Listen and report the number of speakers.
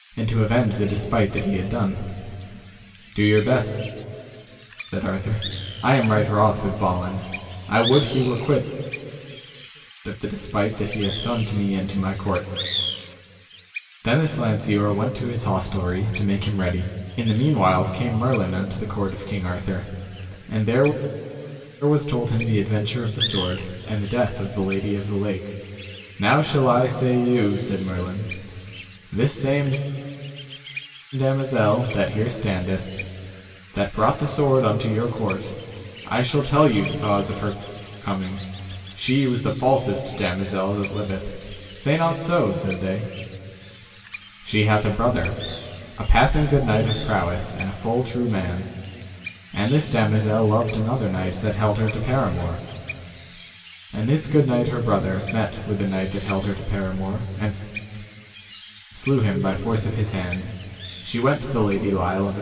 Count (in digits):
1